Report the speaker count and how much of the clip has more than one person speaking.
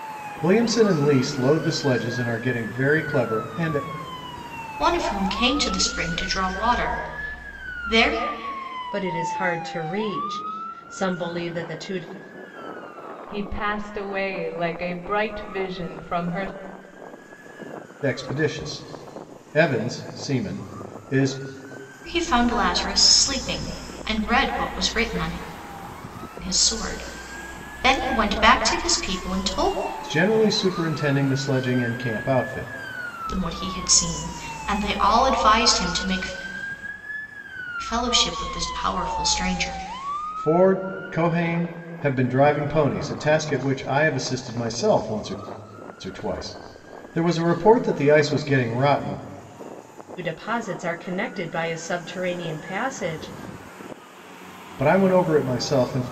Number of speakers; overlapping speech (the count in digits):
4, no overlap